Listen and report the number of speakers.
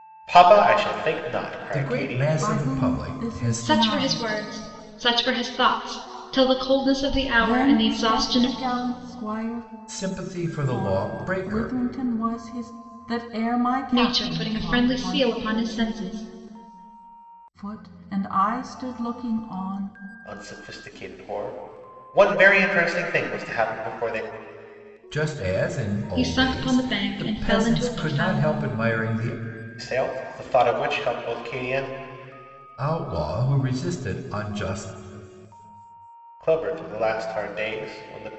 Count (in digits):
4